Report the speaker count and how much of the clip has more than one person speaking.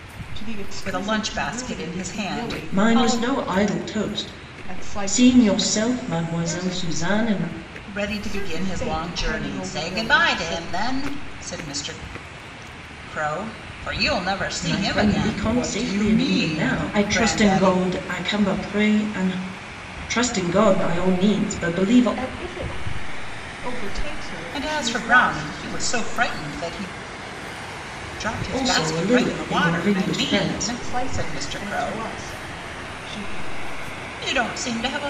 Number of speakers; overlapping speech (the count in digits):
3, about 46%